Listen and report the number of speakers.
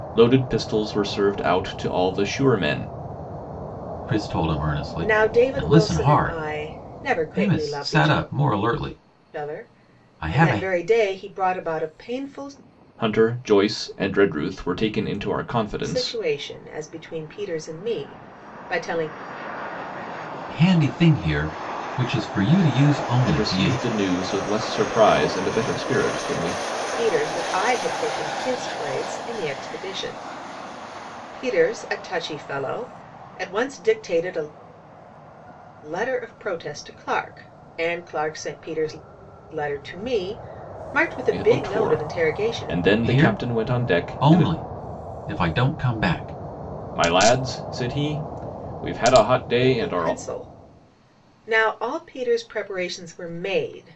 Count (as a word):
three